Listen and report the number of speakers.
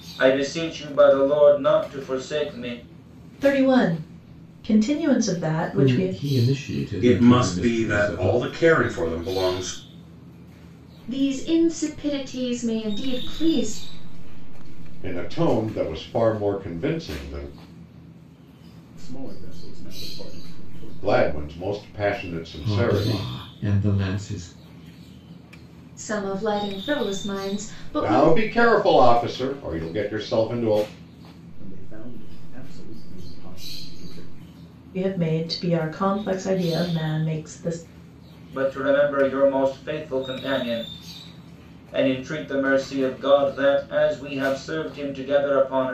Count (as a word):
seven